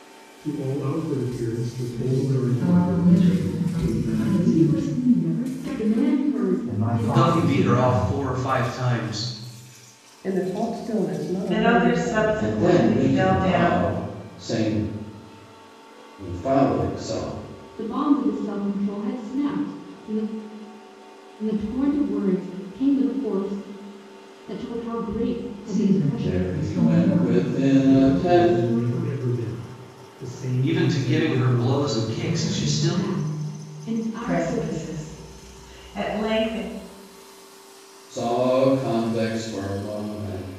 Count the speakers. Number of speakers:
10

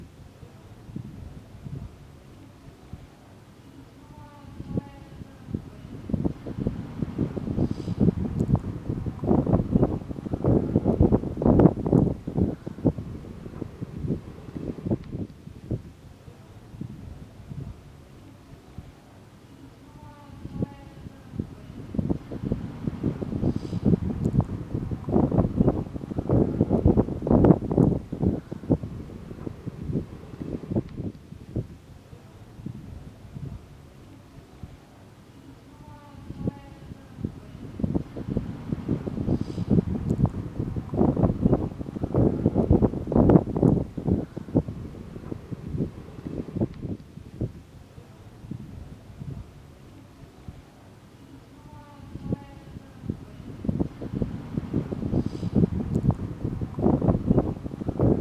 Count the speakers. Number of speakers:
0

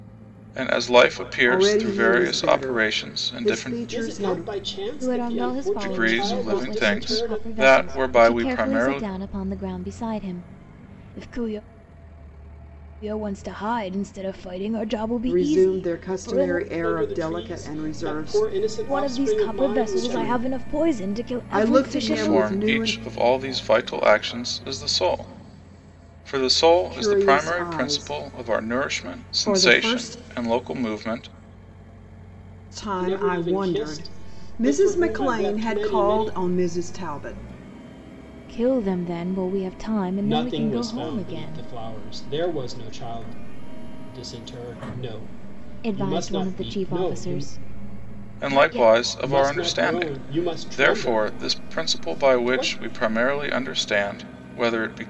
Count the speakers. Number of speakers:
4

